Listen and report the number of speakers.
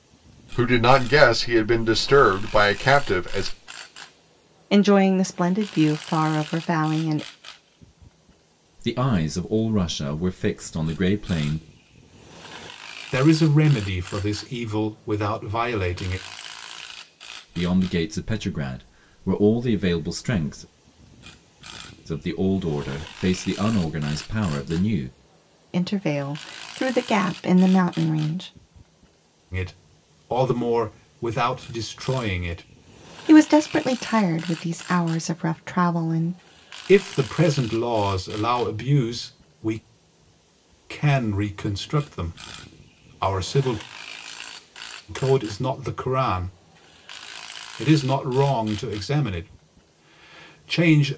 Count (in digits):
4